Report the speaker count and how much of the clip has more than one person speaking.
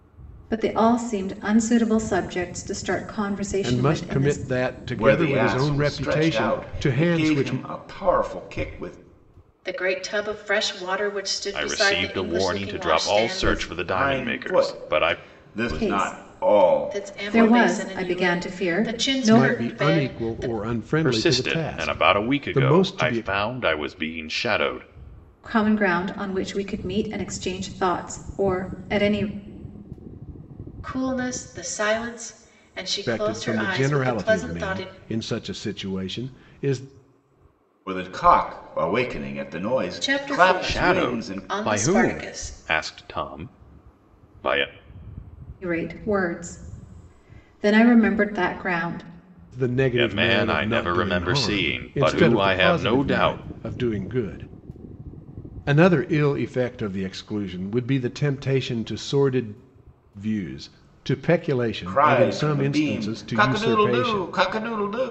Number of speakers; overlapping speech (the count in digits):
5, about 38%